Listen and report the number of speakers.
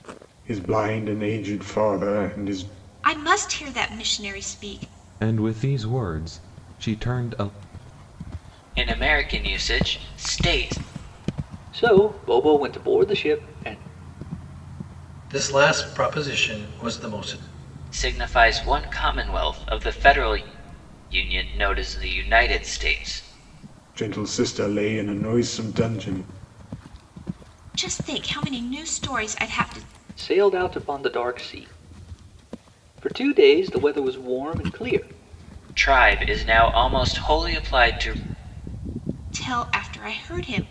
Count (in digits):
6